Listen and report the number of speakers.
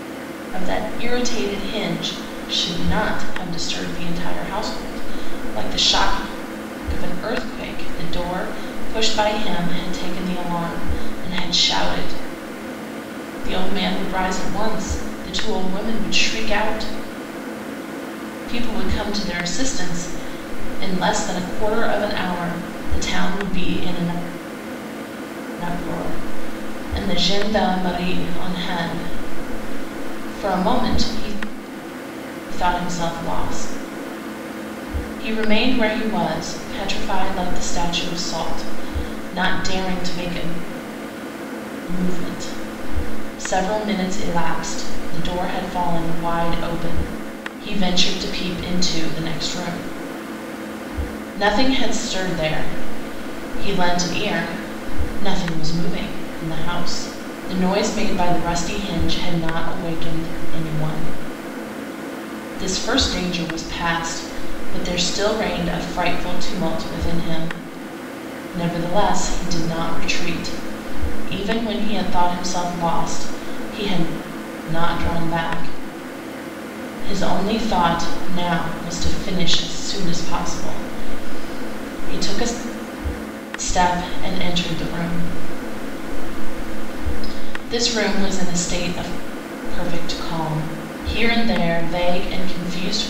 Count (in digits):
1